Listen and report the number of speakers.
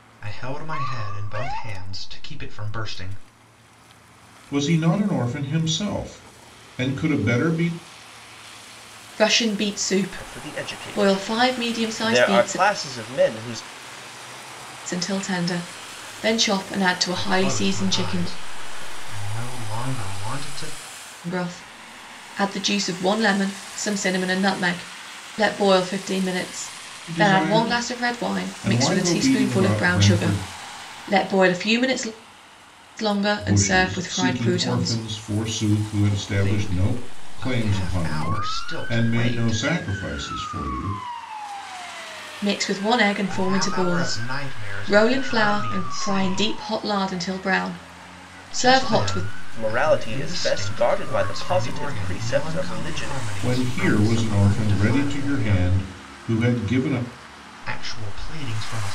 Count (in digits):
4